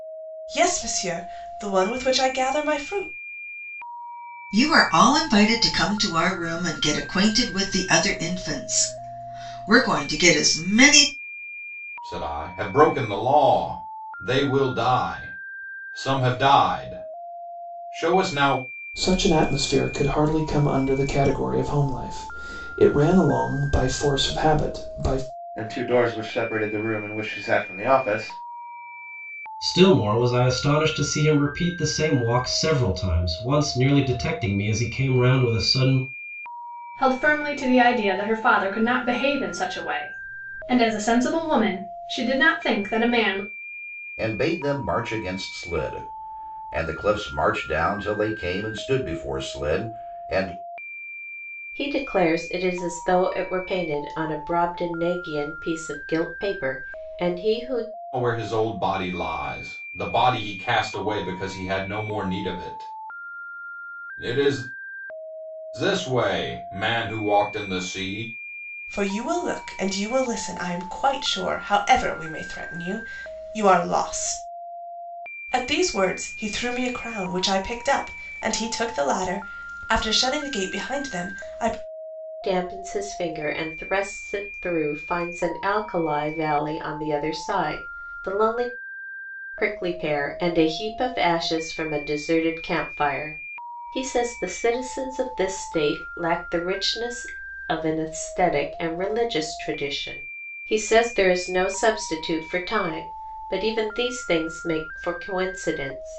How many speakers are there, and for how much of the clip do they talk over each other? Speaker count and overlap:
9, no overlap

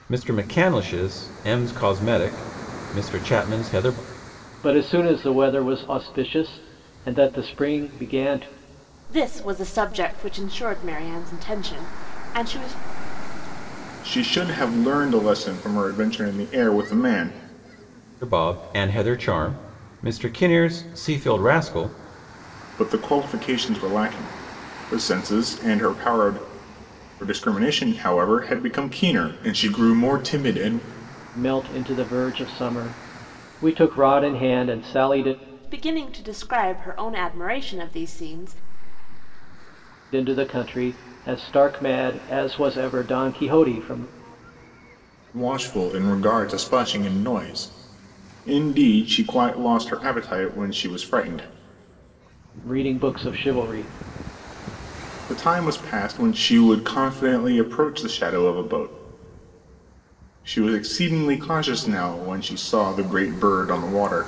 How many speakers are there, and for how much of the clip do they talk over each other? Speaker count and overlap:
4, no overlap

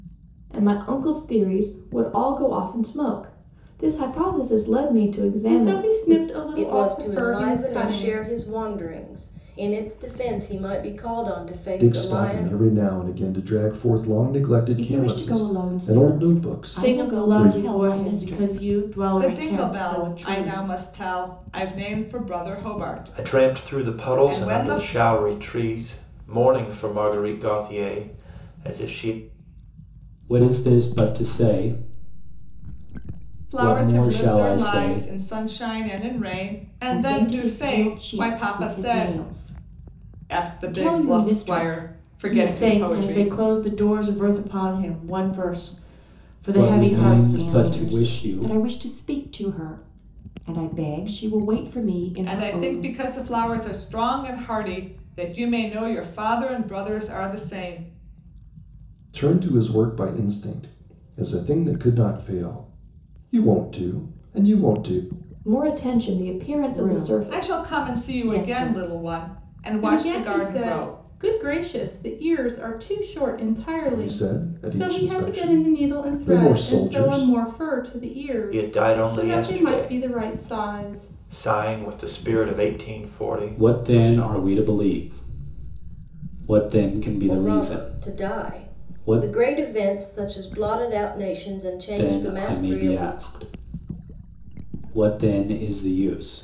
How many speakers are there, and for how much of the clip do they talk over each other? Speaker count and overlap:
9, about 35%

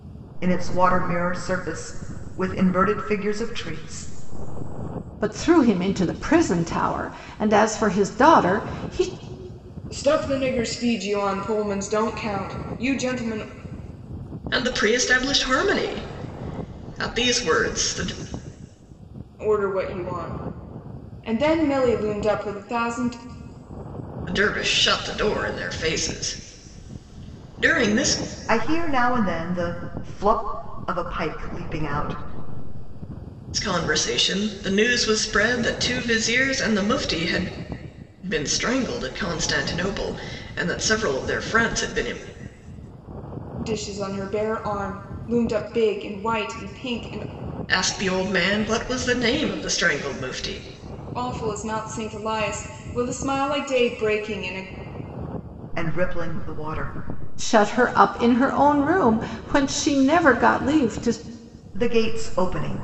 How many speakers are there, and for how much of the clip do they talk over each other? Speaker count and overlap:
4, no overlap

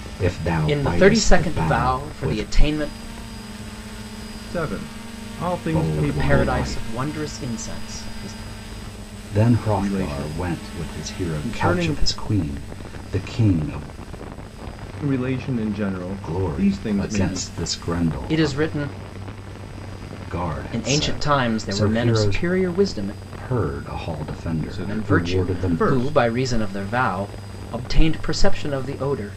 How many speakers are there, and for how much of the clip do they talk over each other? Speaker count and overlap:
3, about 39%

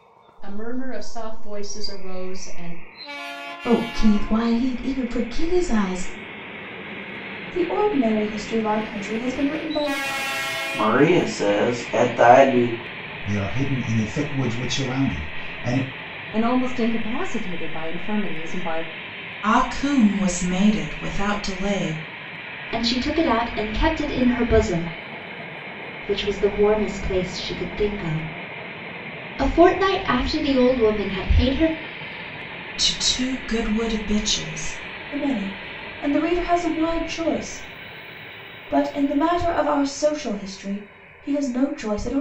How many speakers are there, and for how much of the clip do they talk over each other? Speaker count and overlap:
8, no overlap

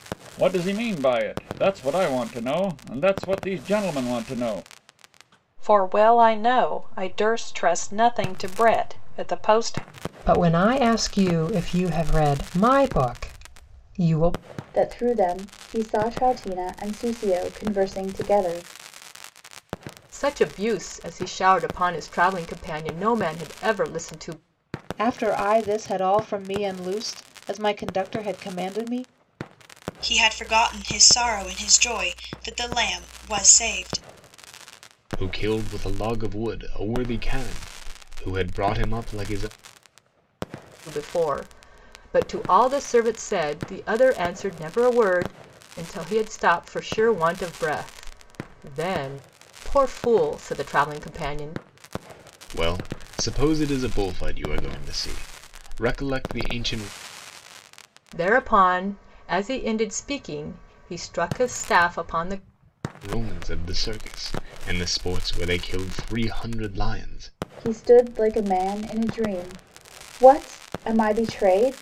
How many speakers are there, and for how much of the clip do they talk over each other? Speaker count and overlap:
8, no overlap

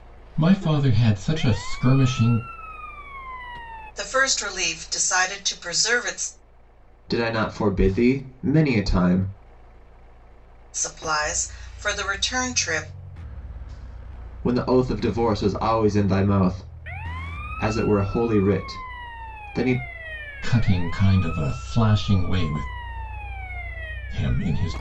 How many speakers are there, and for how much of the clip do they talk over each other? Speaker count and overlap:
3, no overlap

